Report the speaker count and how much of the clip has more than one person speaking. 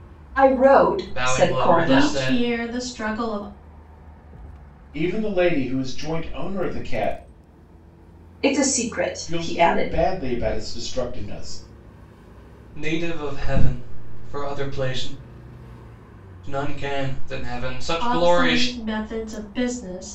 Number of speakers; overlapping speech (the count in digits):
4, about 15%